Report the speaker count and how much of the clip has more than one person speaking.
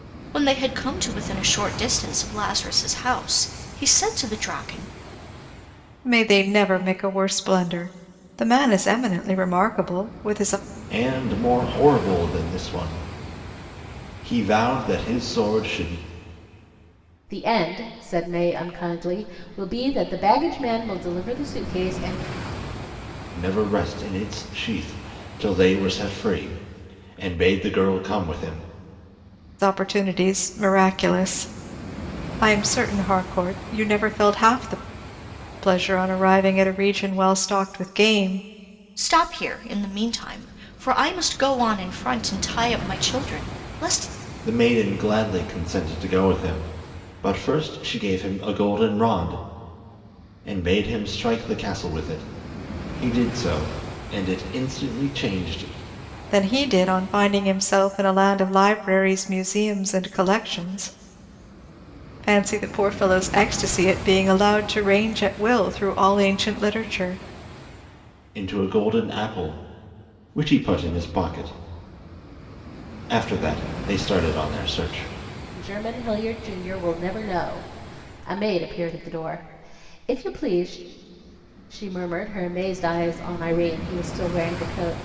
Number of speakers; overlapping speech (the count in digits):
4, no overlap